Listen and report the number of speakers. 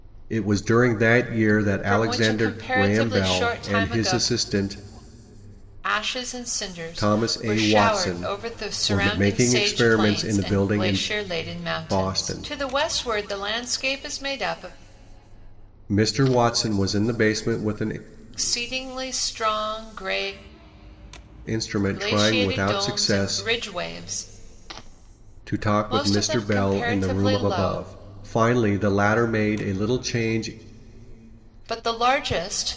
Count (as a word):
two